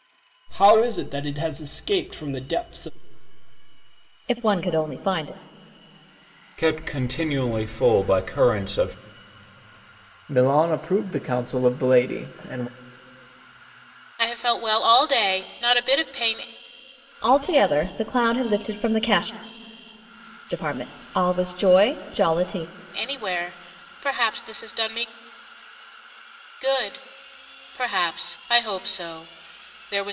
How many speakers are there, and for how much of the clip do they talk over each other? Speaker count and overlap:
five, no overlap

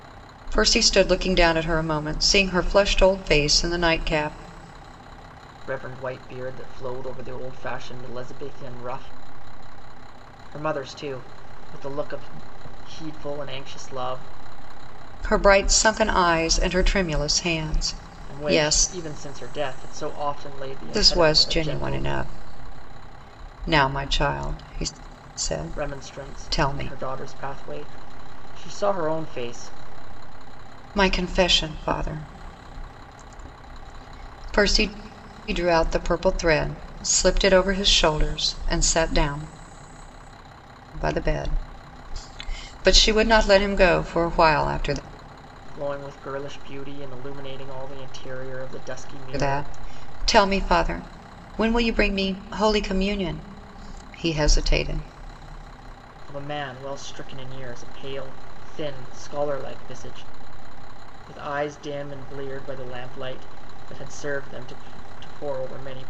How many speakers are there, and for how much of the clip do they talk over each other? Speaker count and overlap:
two, about 5%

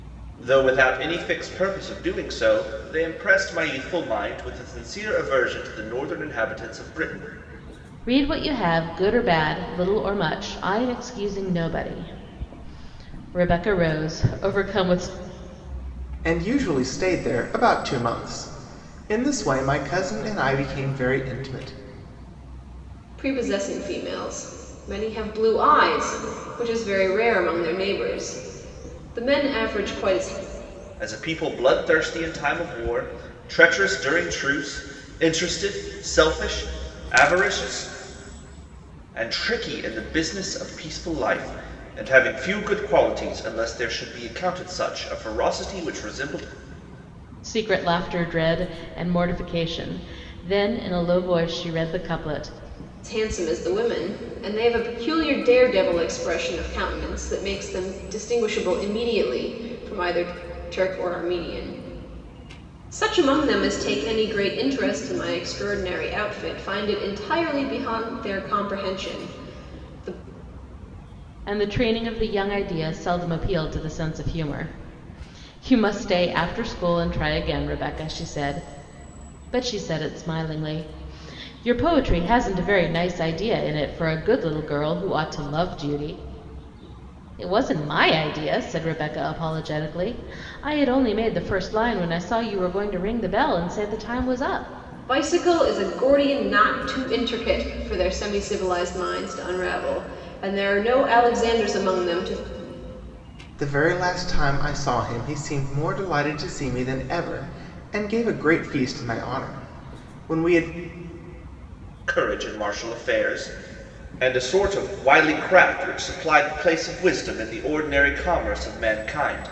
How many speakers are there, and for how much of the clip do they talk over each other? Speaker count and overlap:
four, no overlap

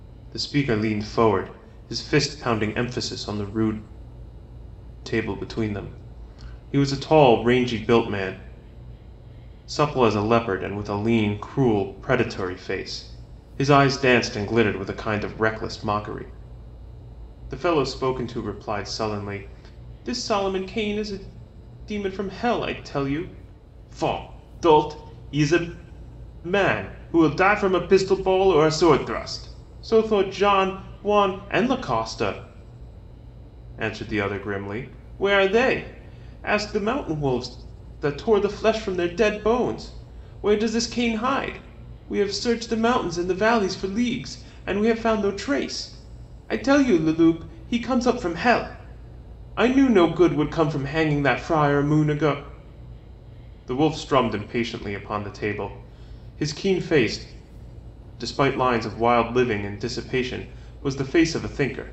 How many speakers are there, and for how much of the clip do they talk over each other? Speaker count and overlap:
one, no overlap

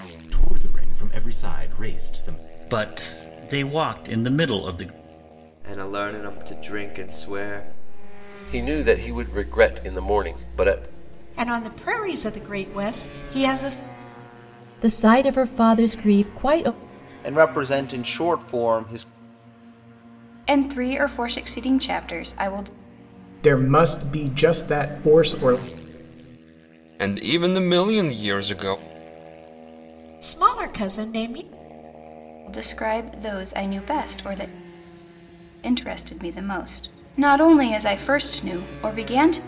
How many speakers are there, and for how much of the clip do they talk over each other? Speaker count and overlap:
ten, no overlap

